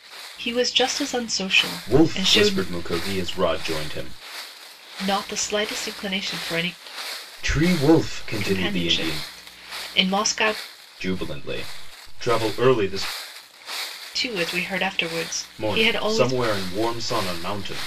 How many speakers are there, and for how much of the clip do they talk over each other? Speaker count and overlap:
two, about 14%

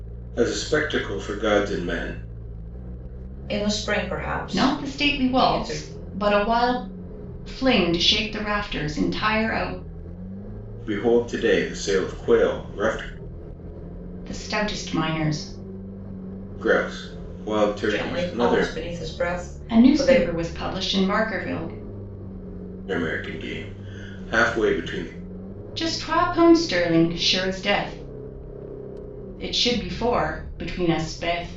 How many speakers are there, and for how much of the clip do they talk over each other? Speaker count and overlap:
three, about 9%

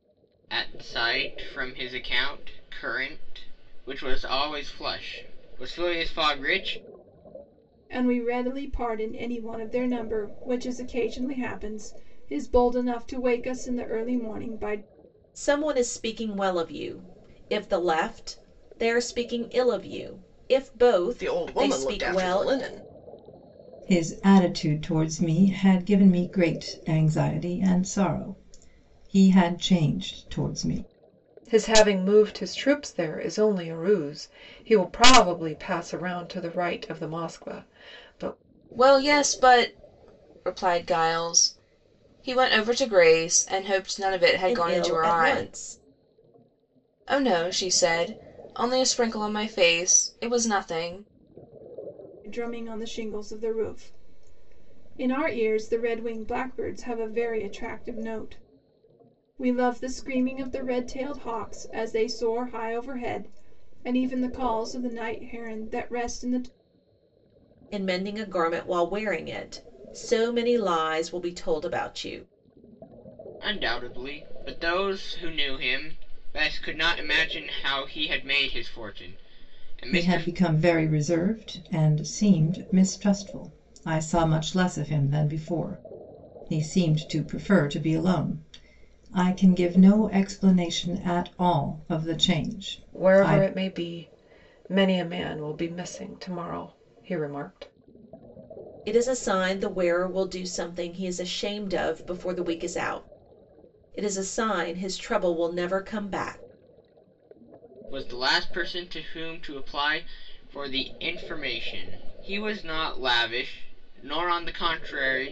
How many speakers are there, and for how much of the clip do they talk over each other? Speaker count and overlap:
seven, about 3%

